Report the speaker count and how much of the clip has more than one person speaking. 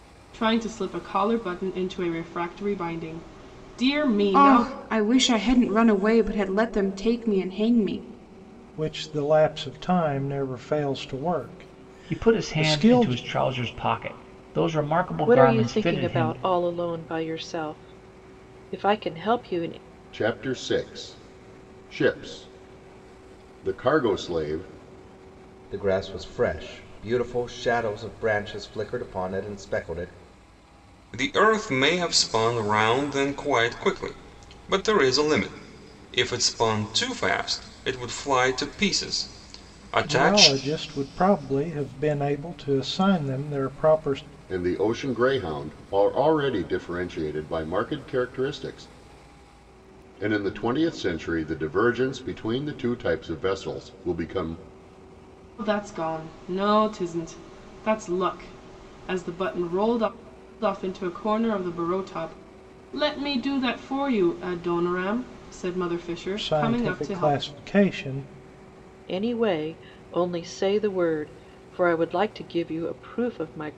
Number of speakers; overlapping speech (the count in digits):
8, about 6%